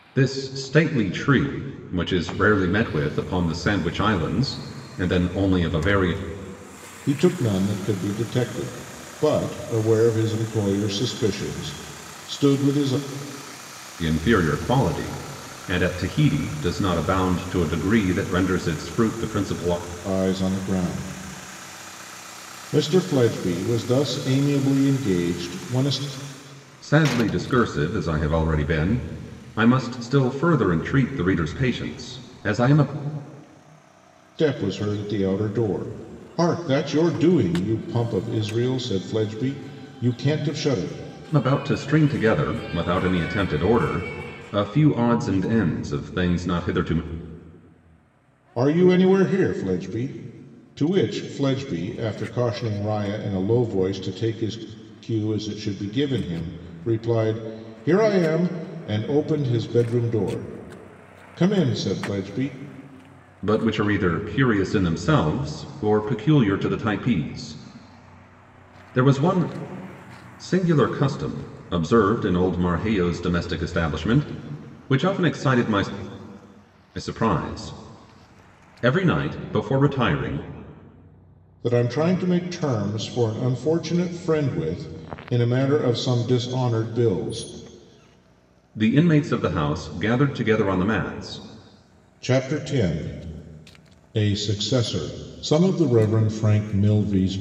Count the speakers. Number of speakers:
two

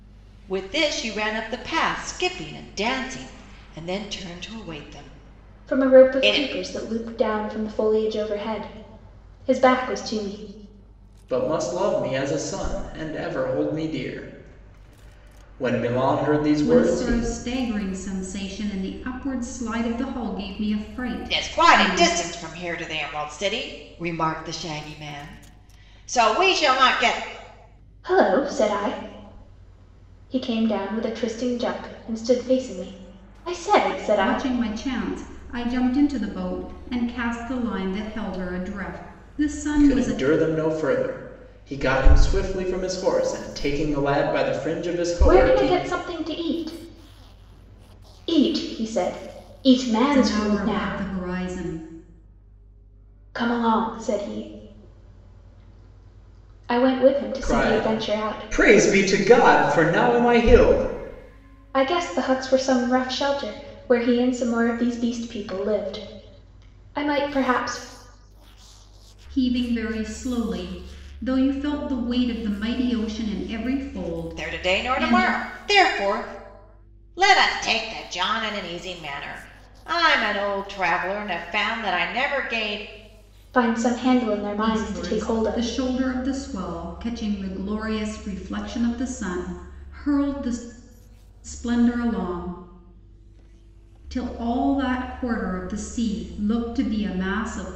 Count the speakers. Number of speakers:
four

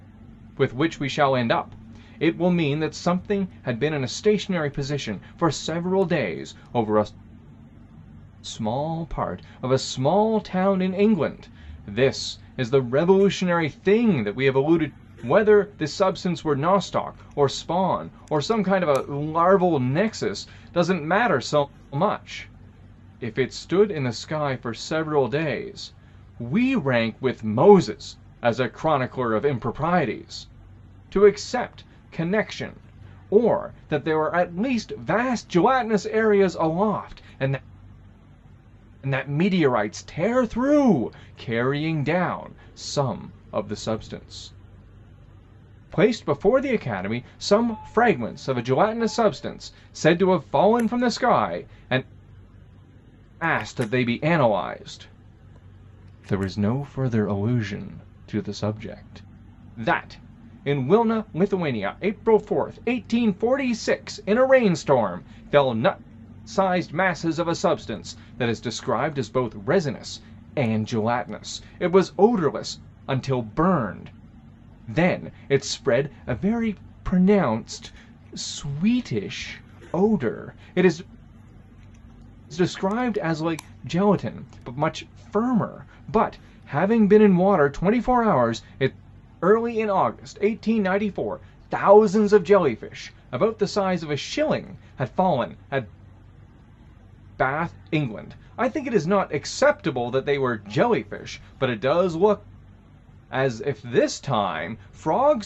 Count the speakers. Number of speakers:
one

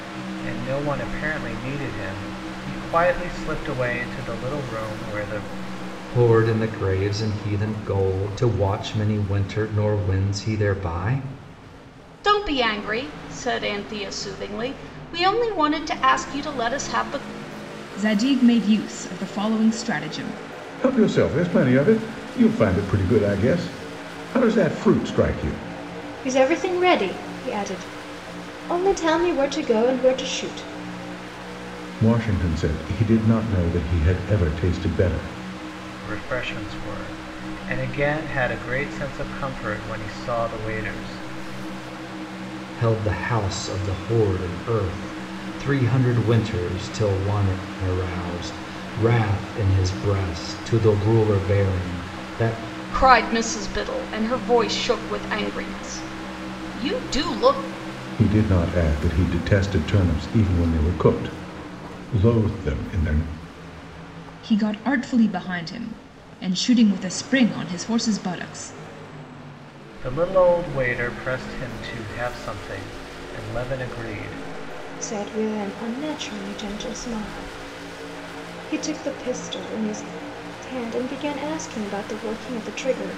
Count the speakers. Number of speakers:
six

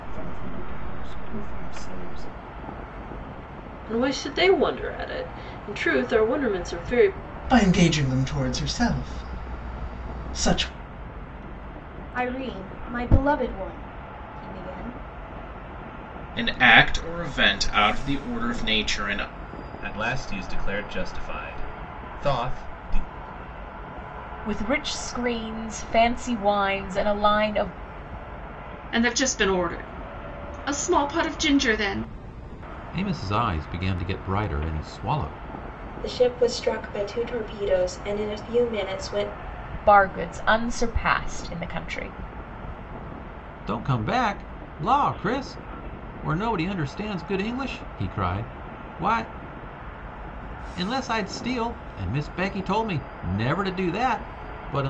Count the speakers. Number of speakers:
ten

